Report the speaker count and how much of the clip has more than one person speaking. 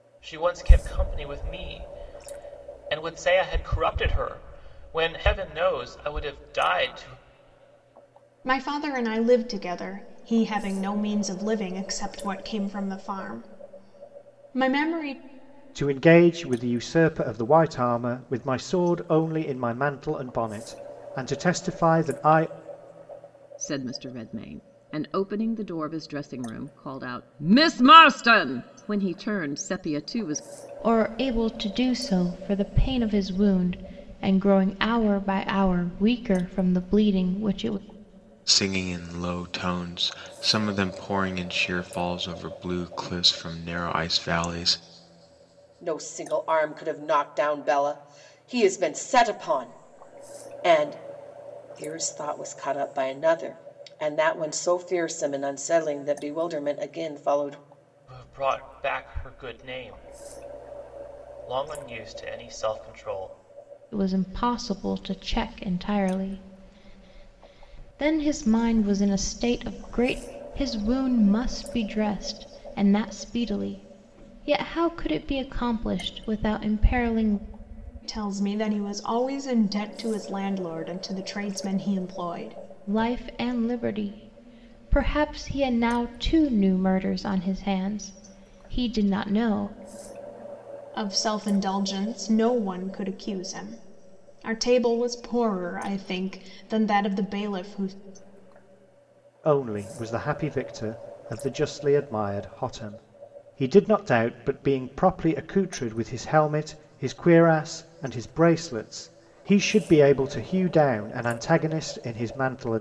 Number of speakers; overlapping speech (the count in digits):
7, no overlap